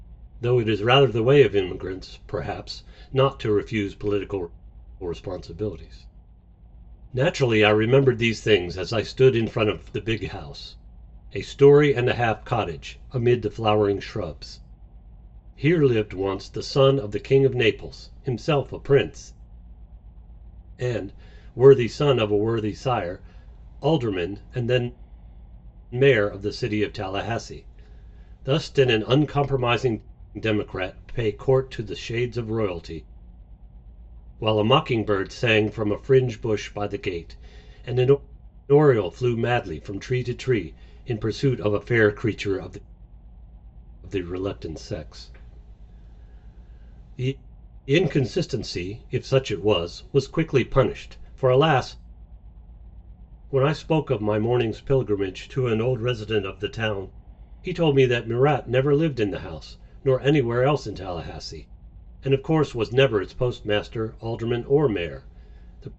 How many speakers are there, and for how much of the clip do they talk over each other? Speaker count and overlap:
1, no overlap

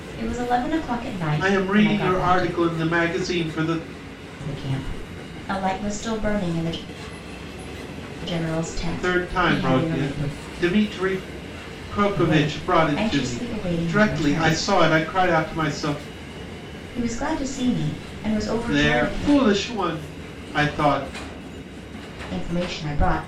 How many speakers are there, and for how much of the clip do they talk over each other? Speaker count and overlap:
2, about 23%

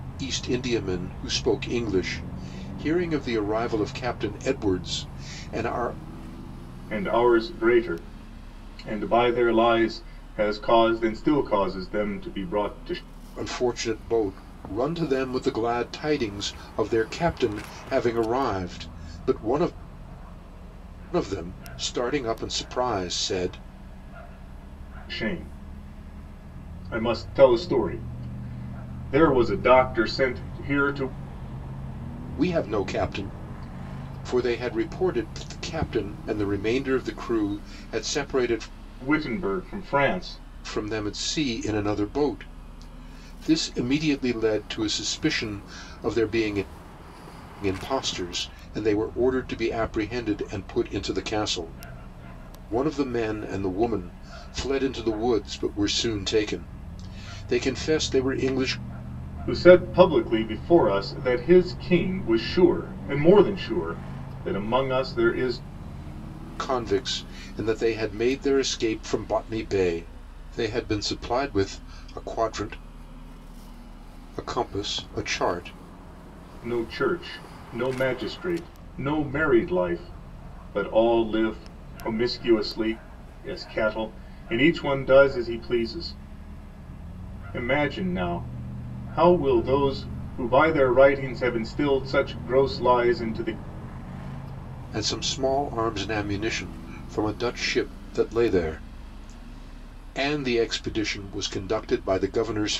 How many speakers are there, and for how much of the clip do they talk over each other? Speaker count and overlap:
2, no overlap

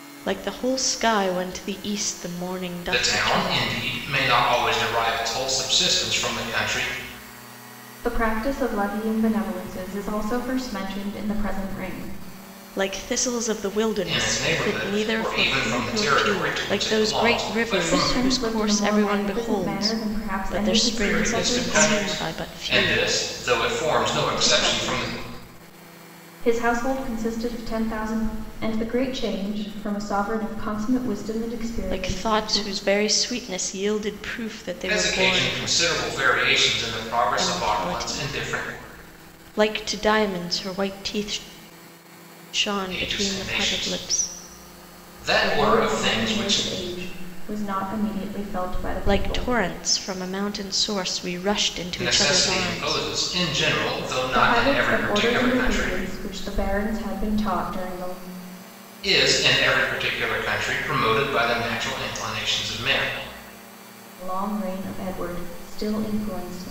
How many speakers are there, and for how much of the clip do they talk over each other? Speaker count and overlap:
3, about 29%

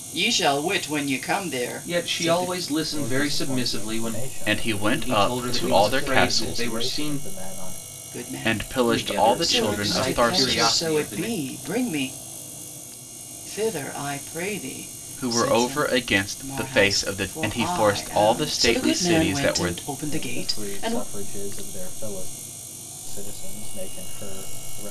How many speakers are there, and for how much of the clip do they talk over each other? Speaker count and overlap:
4, about 52%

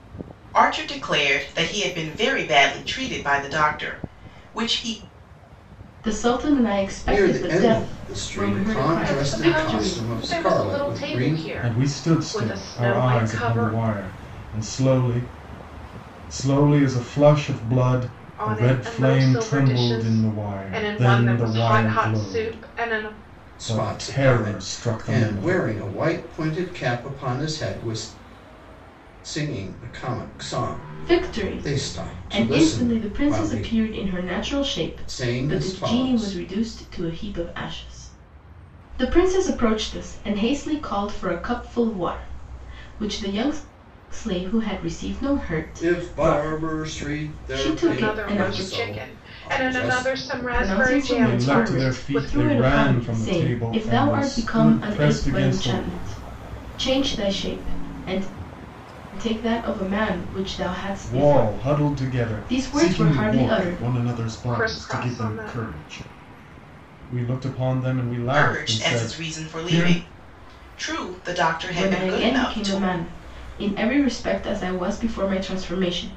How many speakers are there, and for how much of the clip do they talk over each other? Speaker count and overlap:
5, about 44%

